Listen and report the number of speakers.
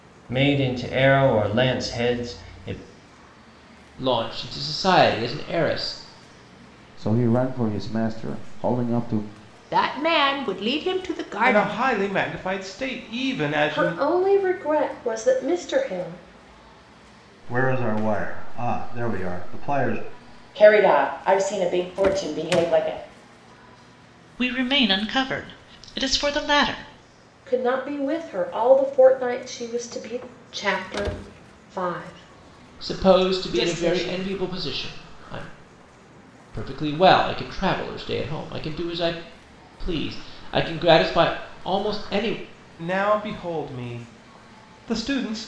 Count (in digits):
9